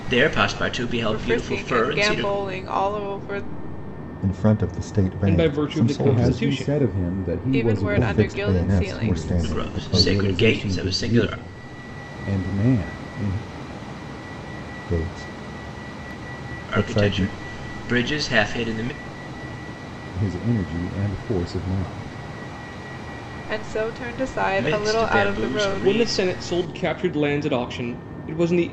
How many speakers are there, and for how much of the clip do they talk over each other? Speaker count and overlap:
5, about 32%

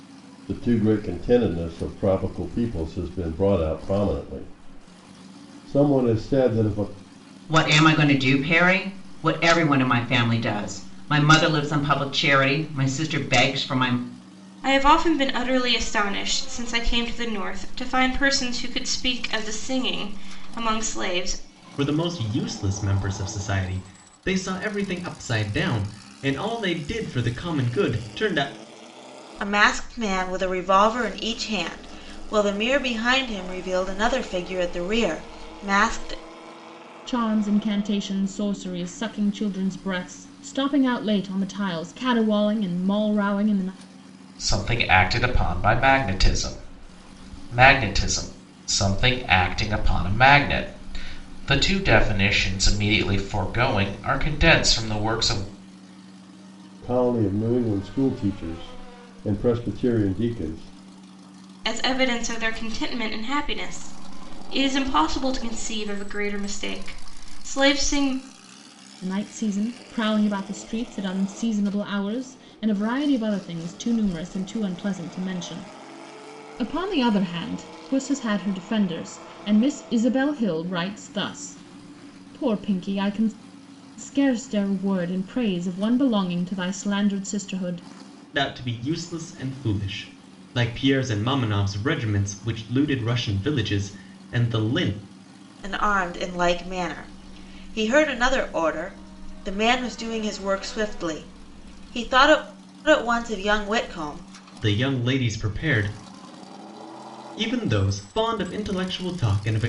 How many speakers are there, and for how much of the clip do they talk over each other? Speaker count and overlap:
7, no overlap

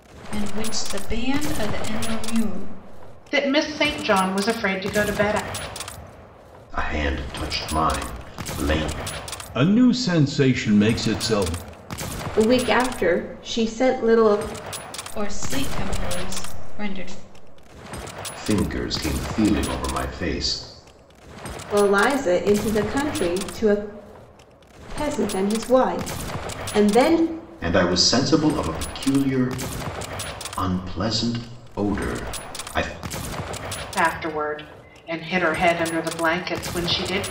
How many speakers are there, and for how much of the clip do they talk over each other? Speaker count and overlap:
5, no overlap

